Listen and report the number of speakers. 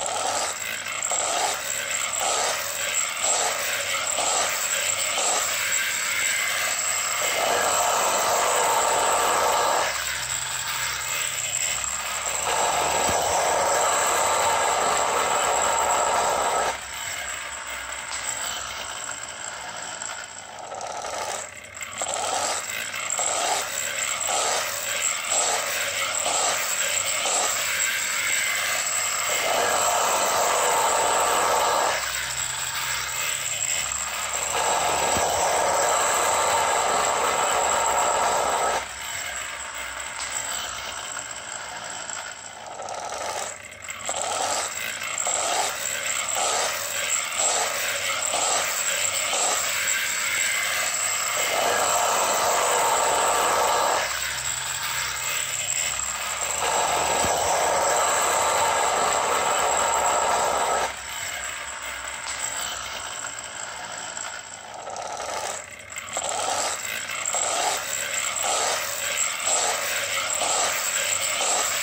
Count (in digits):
0